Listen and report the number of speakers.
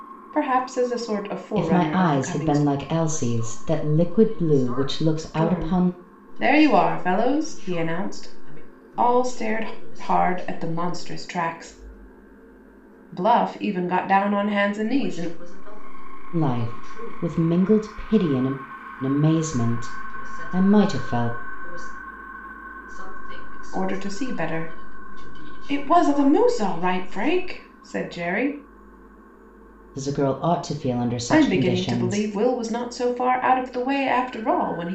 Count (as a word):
three